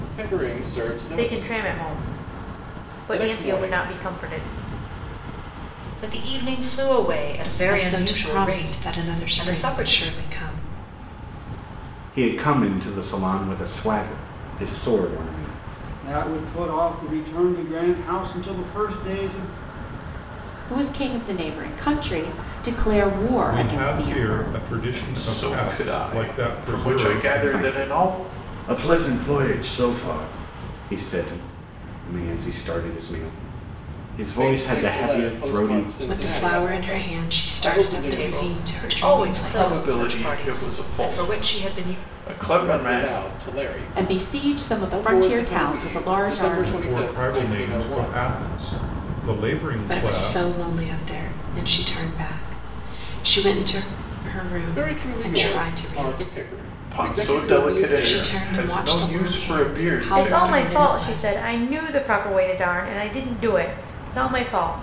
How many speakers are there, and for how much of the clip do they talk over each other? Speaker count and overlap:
9, about 45%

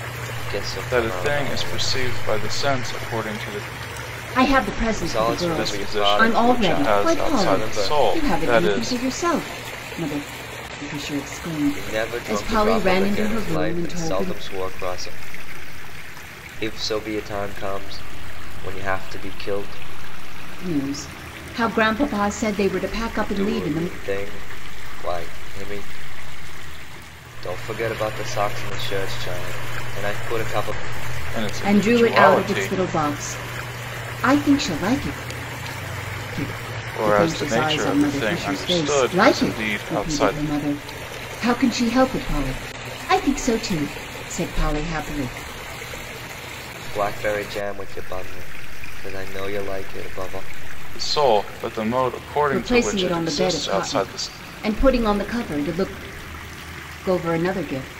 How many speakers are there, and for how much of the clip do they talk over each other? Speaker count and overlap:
3, about 26%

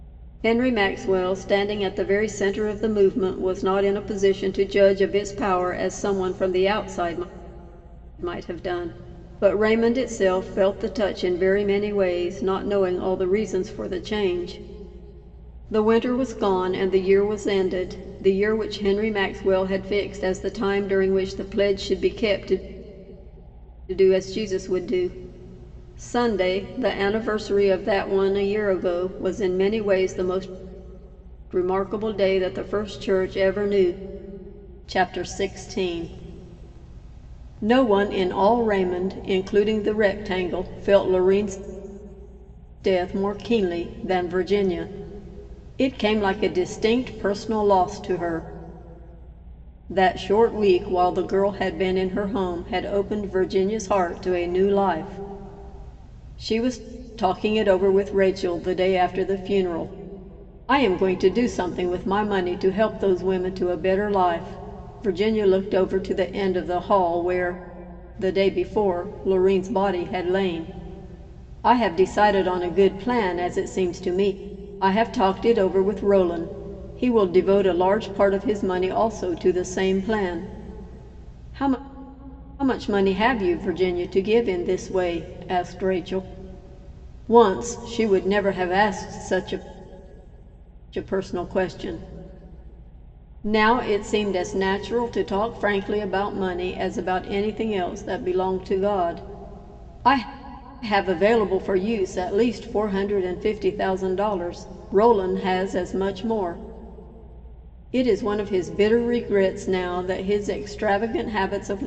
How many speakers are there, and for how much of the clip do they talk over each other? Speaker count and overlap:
1, no overlap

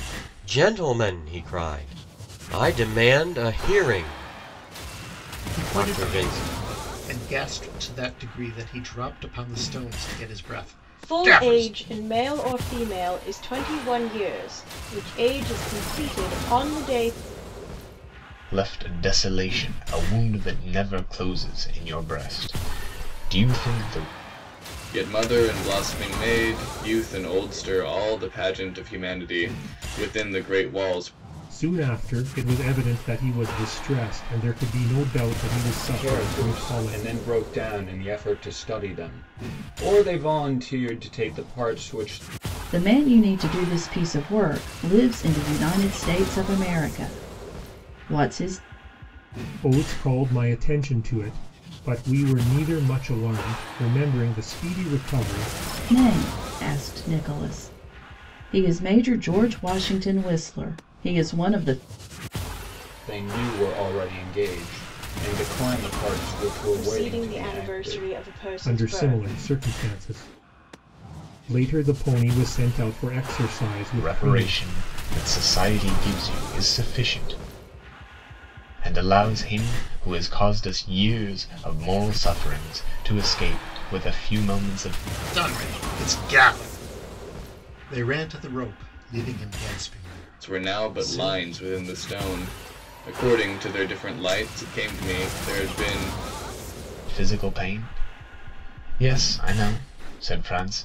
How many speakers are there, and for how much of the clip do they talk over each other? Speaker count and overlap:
8, about 7%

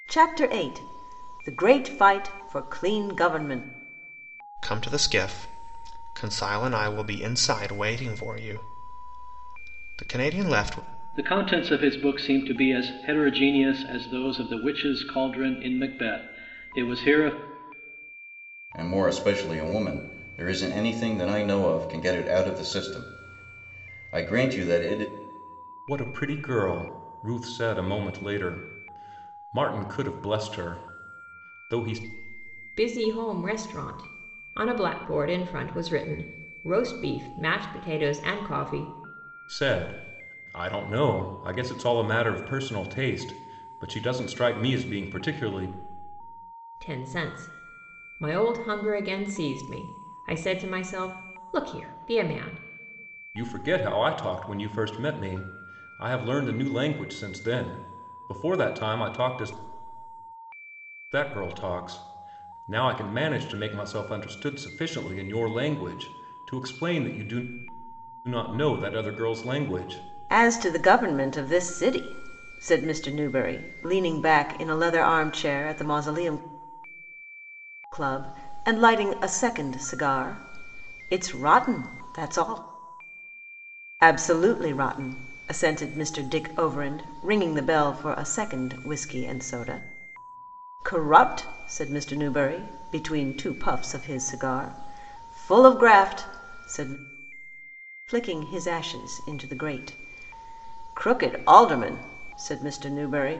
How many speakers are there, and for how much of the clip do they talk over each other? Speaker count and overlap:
6, no overlap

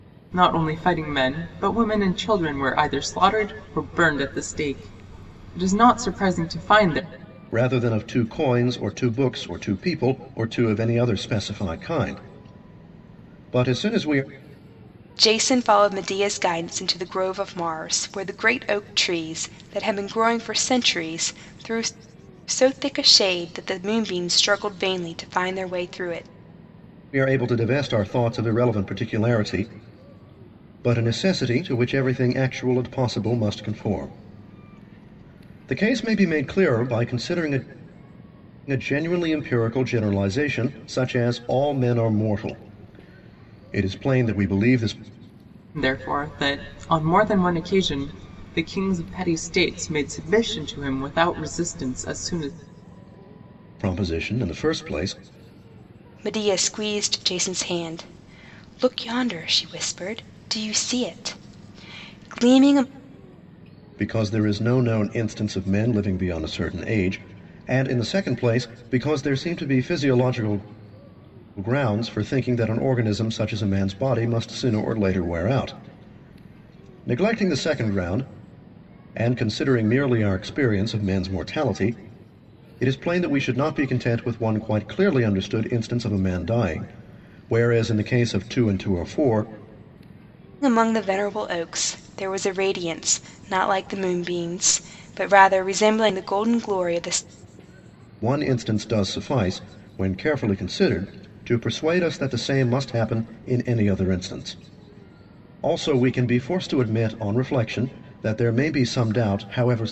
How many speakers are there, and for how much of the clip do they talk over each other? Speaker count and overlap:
3, no overlap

